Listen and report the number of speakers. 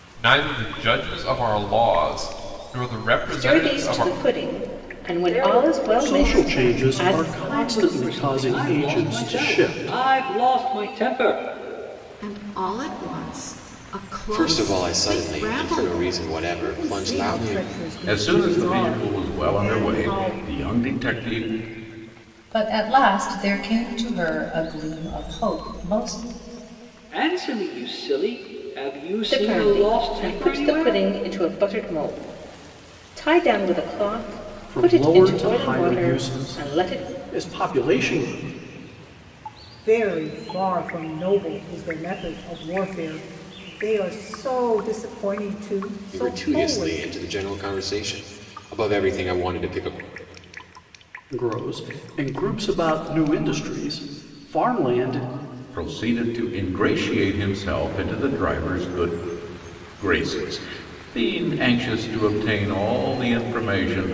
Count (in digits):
10